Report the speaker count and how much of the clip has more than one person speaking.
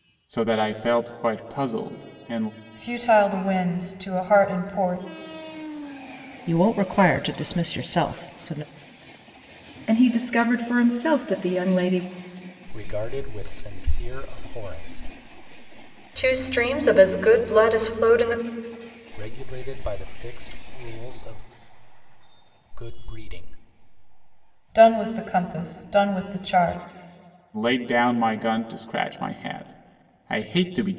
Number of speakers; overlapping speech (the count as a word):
six, no overlap